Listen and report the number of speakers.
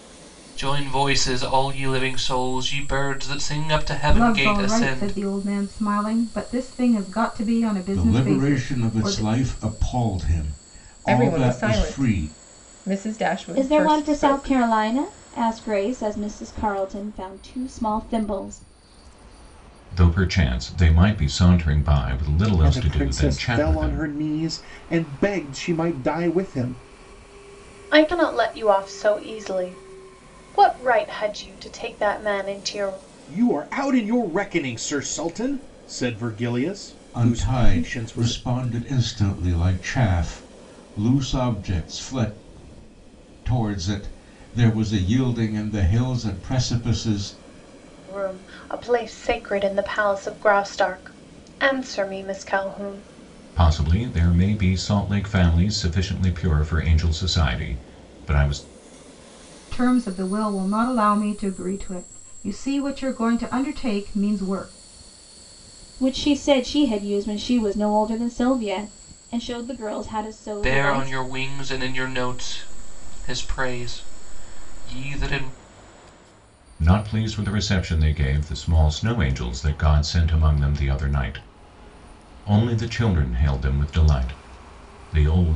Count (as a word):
eight